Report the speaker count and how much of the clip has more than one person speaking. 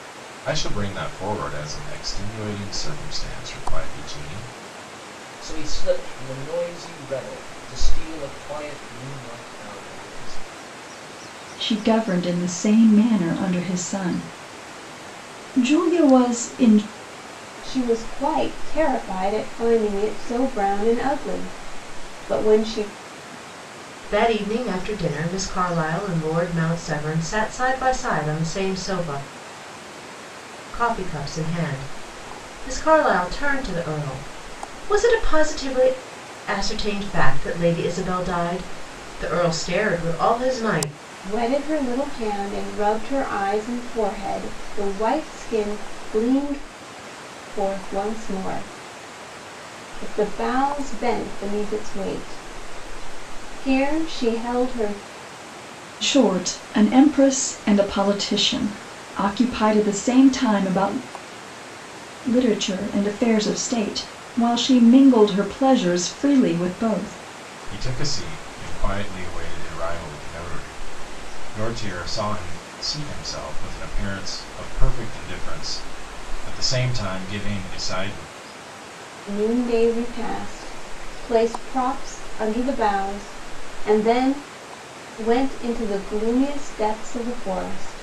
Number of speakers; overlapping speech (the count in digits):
5, no overlap